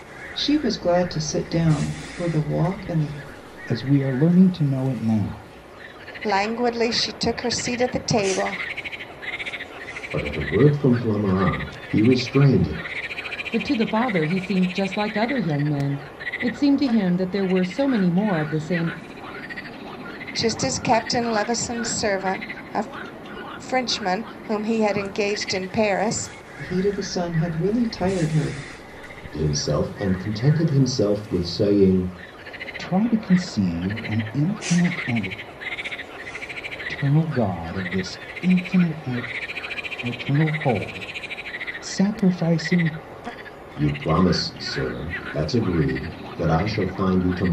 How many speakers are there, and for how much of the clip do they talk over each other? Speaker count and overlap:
five, no overlap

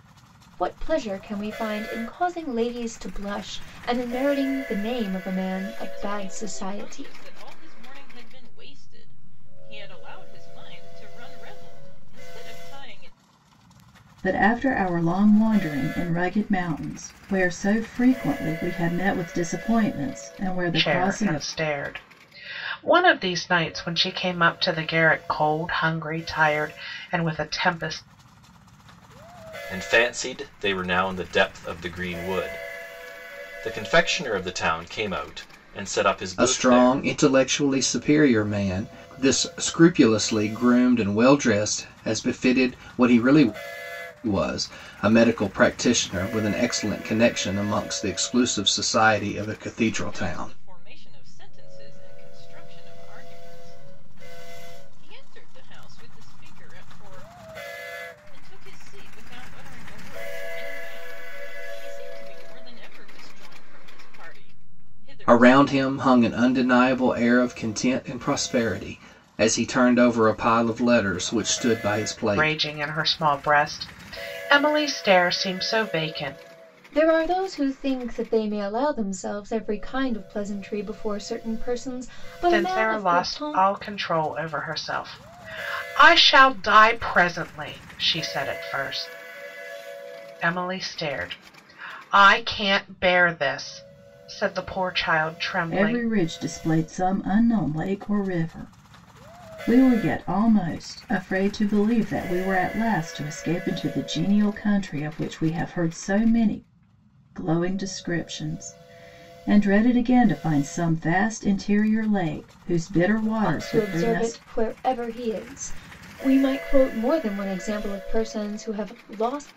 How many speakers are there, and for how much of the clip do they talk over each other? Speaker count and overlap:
six, about 6%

